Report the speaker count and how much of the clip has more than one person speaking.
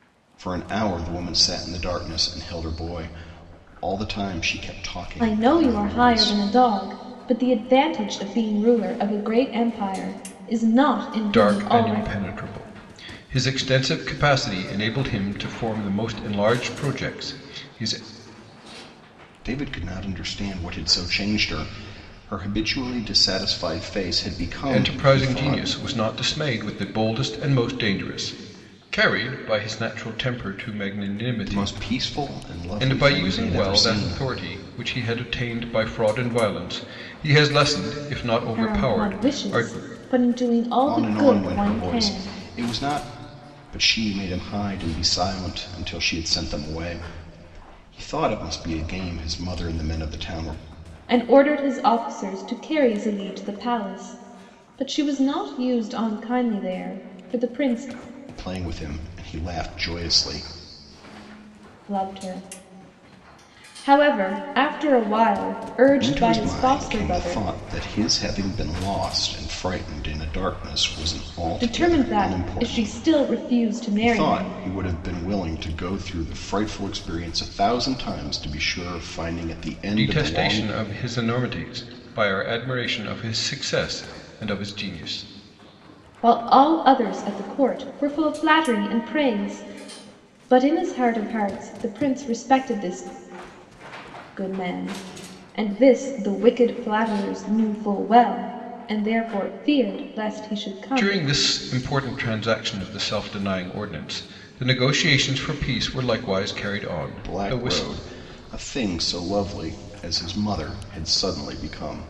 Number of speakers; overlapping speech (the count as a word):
three, about 11%